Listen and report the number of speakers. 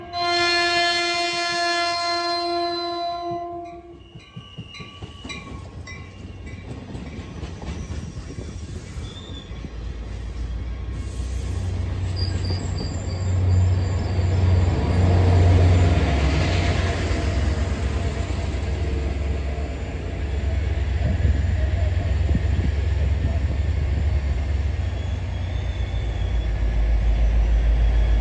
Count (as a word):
zero